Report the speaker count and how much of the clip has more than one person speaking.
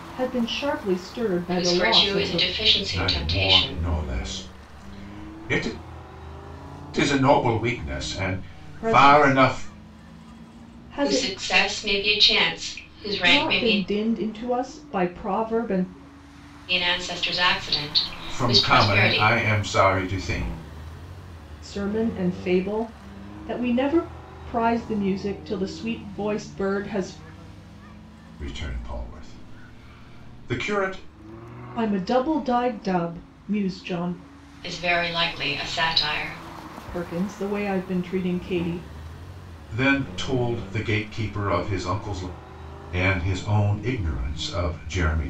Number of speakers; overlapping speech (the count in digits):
3, about 11%